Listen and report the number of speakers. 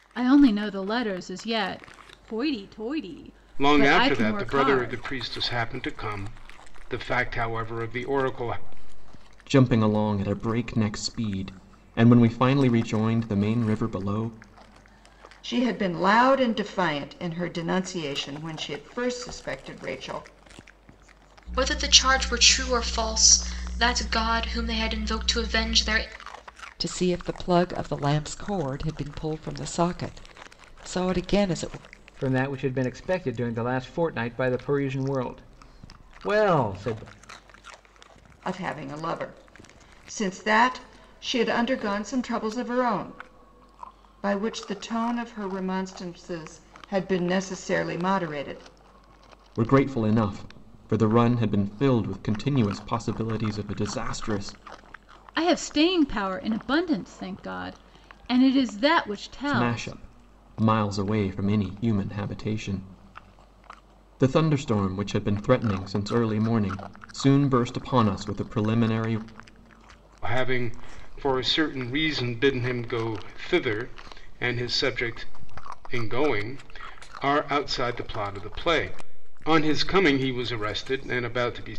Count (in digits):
7